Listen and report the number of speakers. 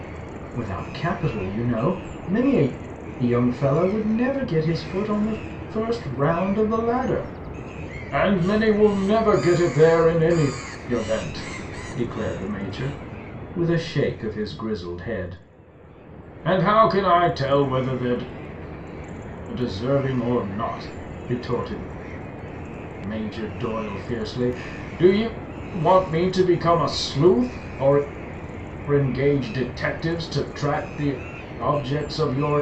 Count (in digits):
1